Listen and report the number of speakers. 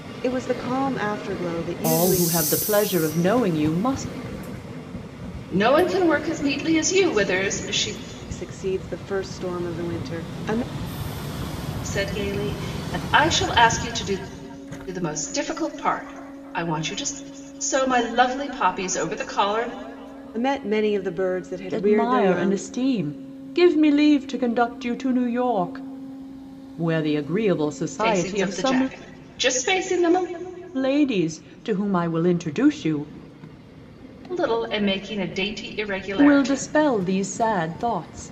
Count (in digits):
3